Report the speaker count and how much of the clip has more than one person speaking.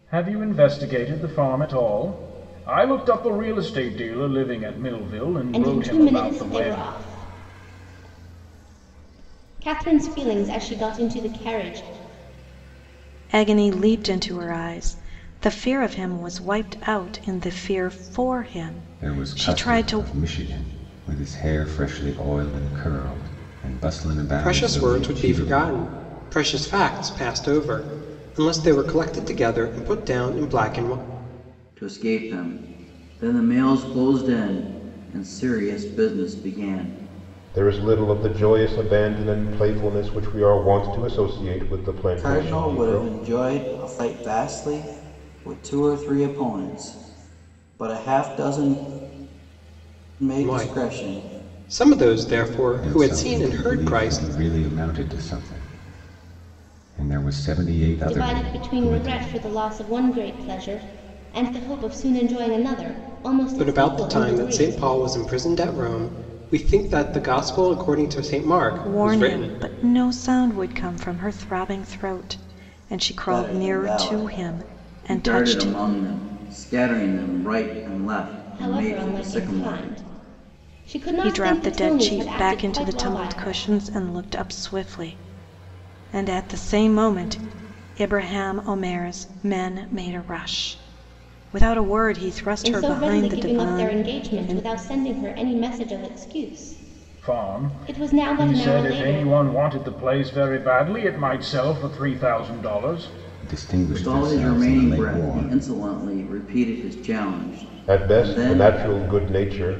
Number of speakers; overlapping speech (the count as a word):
seven, about 22%